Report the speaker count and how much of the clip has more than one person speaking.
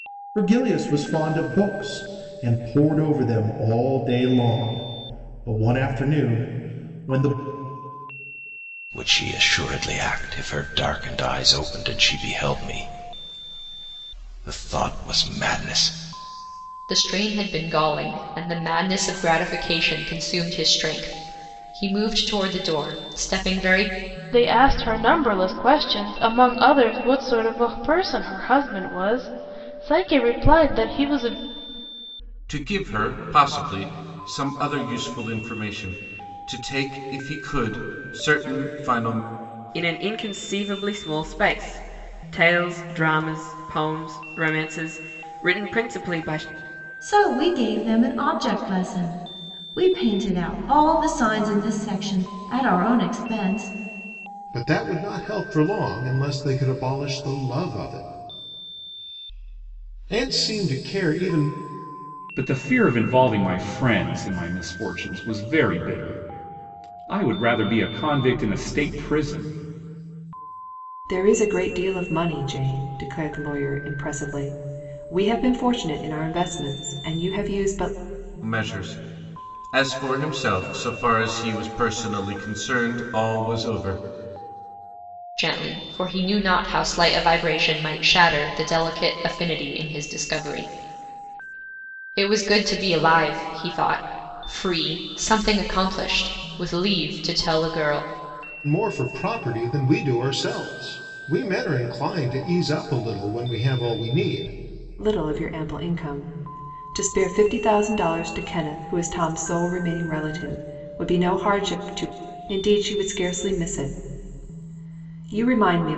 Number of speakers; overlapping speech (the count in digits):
10, no overlap